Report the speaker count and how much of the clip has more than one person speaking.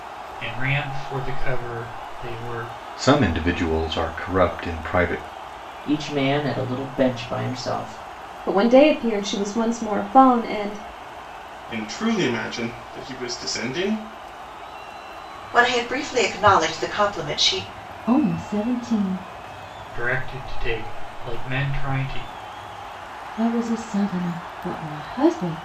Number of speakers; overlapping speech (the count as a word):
seven, no overlap